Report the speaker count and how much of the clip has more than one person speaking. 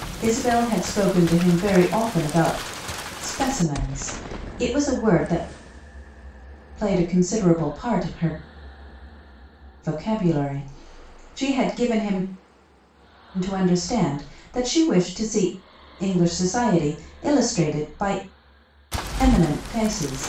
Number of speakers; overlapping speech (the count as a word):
one, no overlap